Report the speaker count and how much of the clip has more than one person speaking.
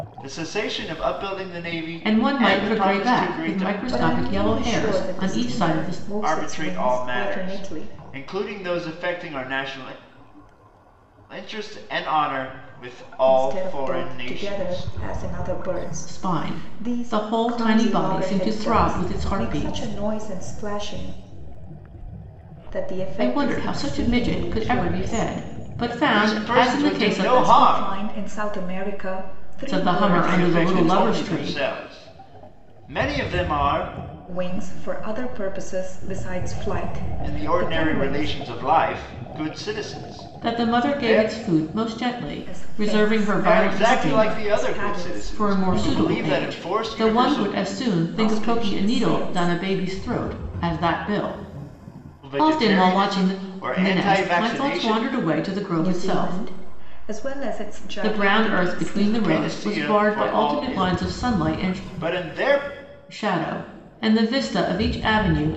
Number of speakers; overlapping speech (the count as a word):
three, about 50%